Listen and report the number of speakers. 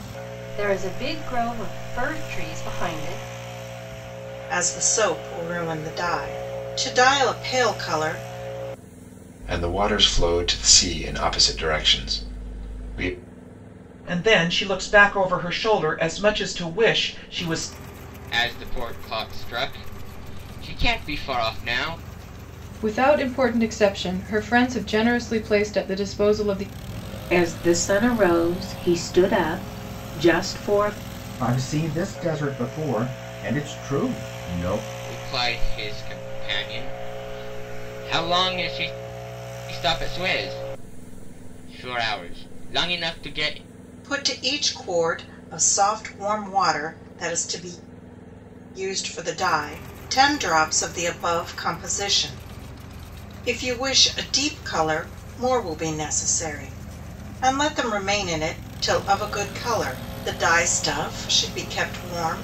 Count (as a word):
eight